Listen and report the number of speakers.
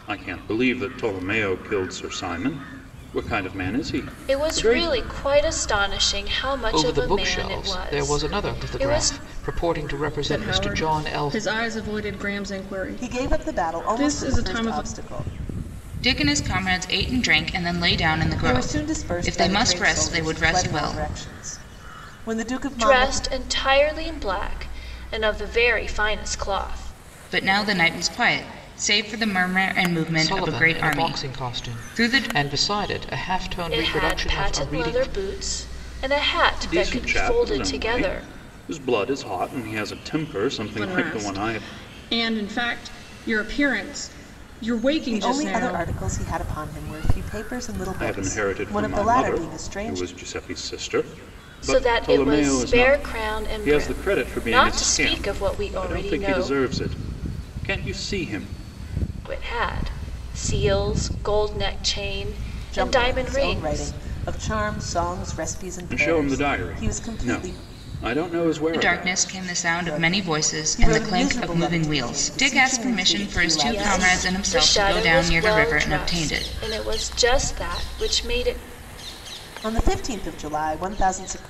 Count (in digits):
6